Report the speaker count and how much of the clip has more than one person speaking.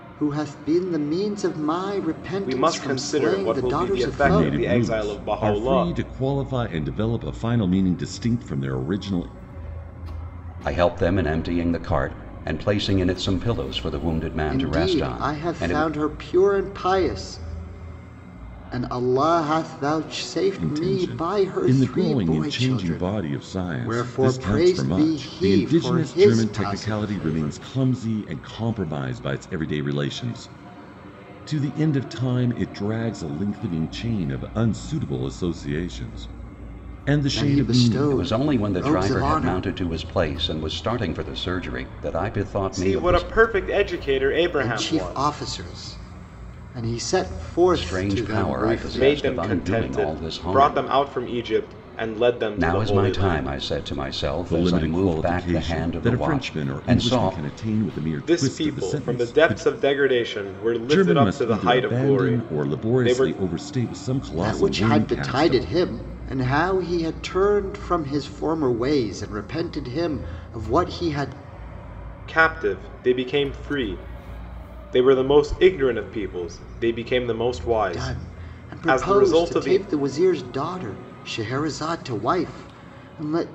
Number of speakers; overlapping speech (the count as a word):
four, about 35%